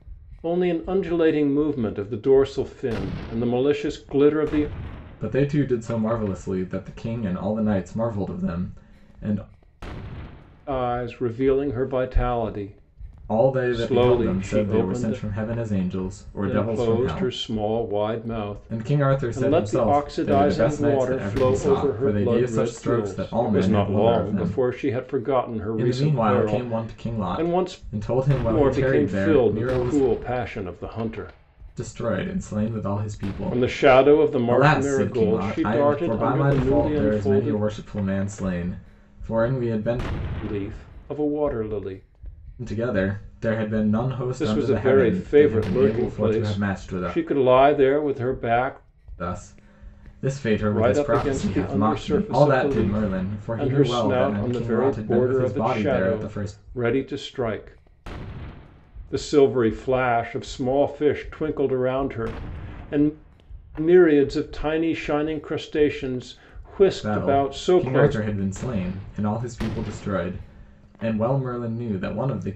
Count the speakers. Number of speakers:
2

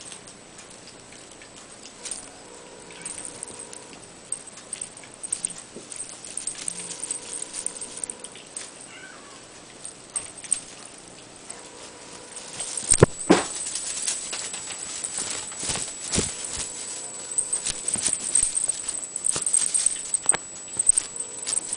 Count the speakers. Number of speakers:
0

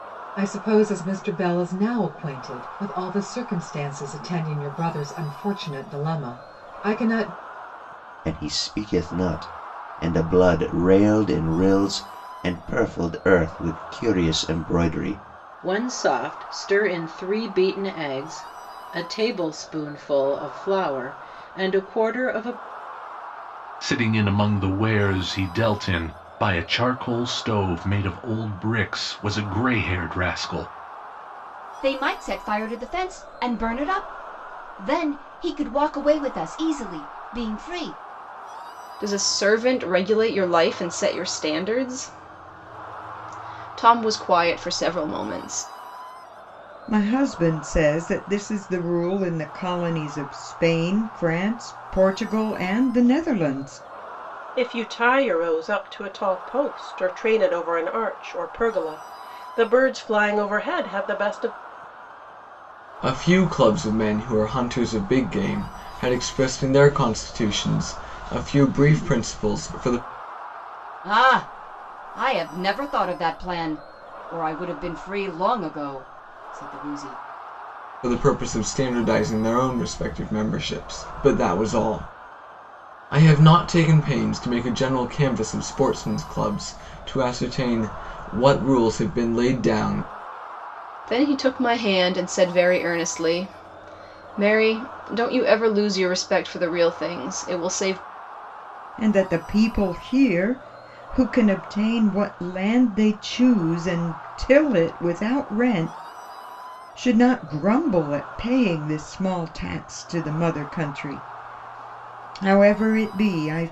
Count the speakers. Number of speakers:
9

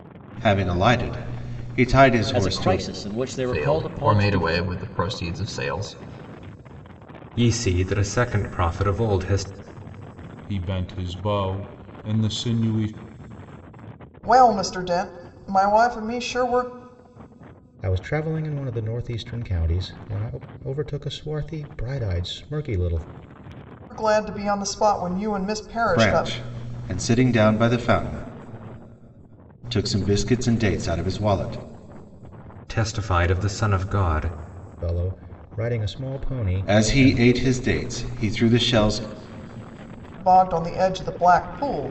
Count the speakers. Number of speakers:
7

